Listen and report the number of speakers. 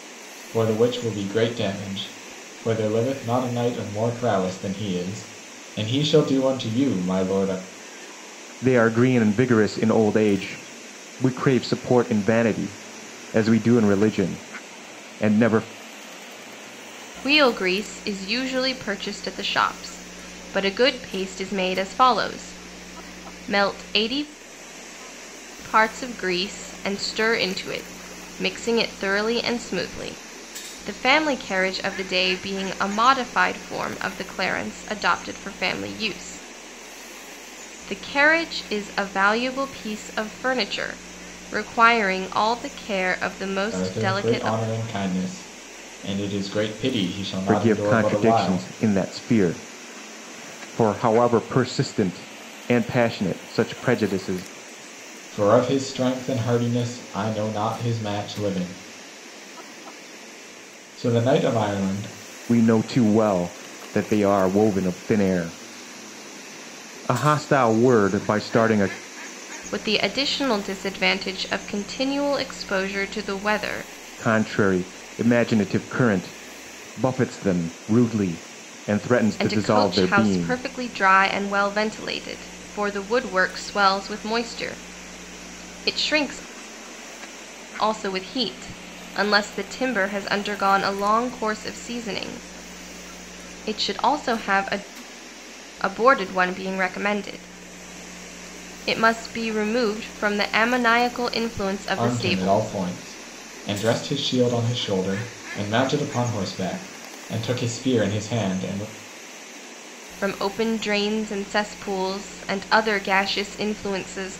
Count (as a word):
three